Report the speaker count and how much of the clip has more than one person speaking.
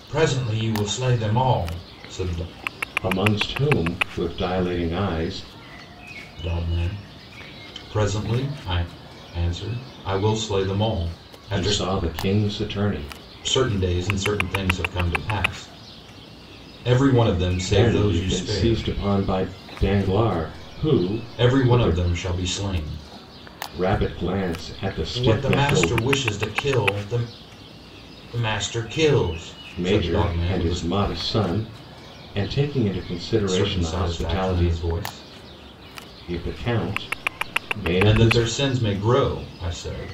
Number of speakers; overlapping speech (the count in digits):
2, about 15%